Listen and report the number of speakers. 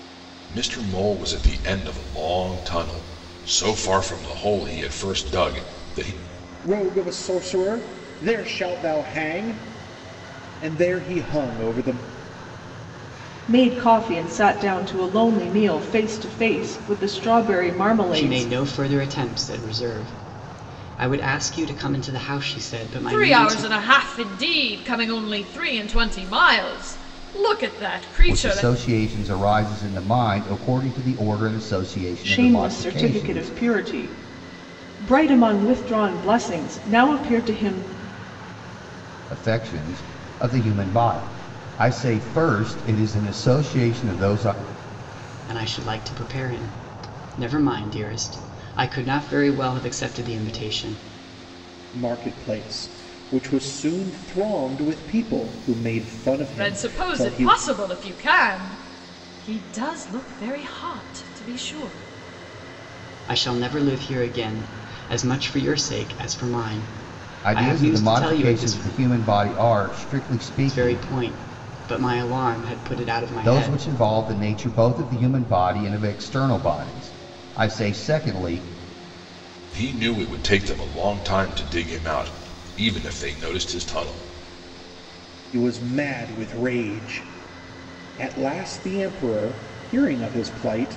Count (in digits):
6